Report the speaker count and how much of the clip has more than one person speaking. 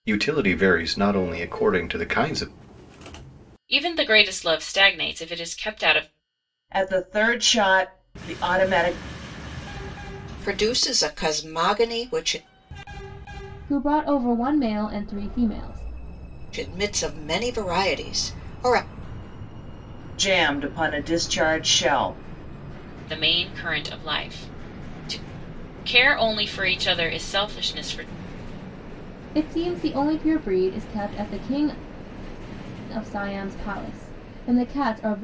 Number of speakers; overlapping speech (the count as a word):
five, no overlap